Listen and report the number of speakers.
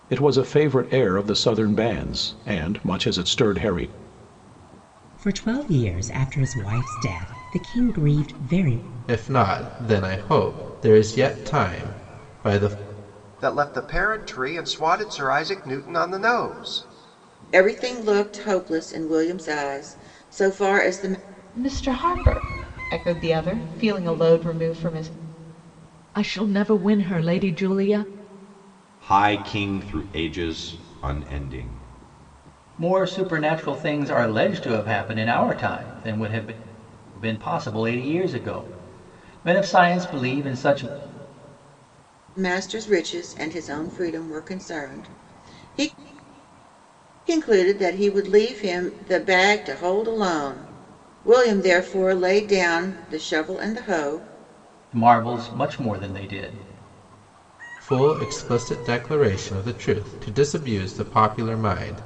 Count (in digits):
9